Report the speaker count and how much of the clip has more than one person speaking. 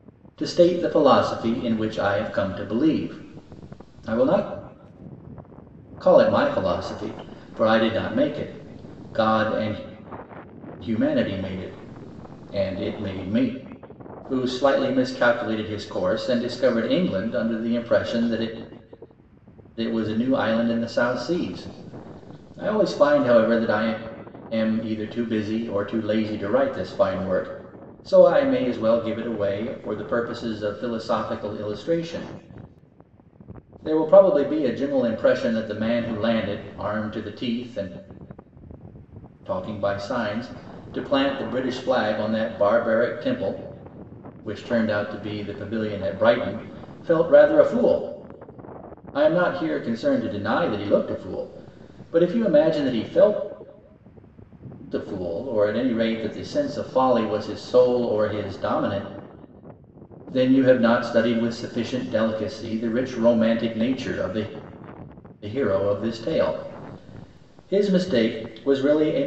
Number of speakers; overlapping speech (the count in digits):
1, no overlap